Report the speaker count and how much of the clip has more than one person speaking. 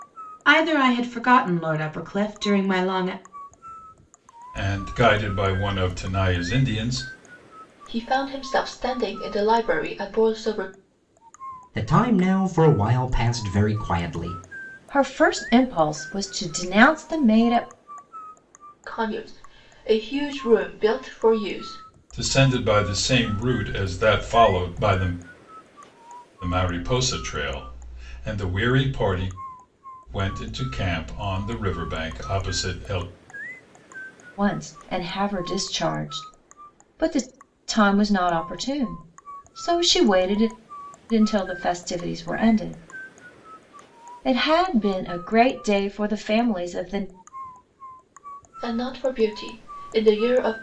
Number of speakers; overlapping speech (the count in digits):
5, no overlap